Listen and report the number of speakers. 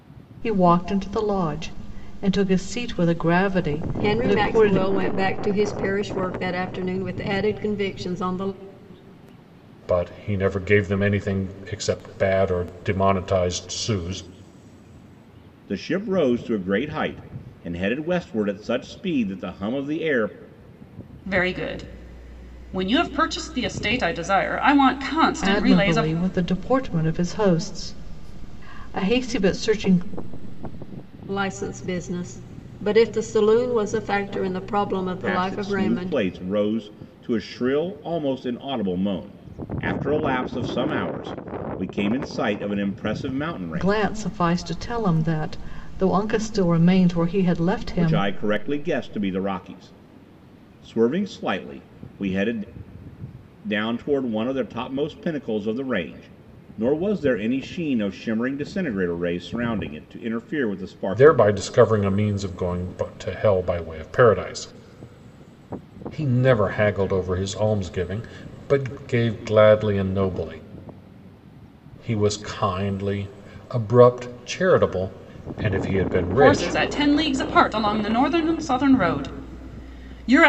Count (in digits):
5